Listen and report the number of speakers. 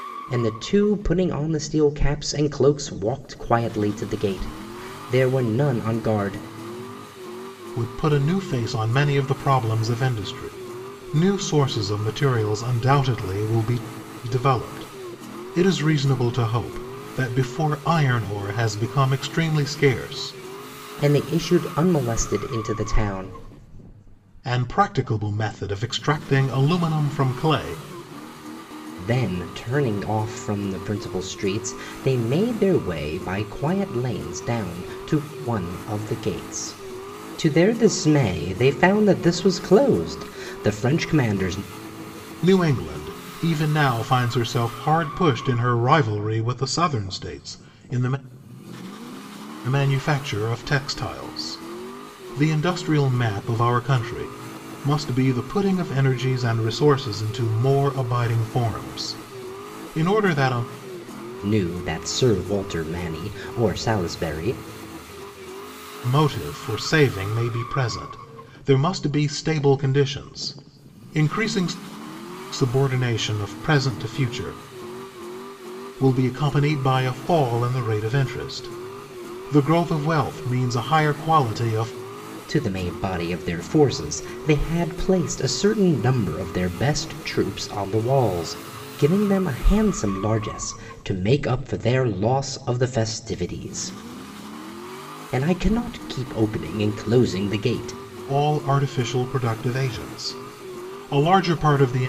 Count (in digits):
2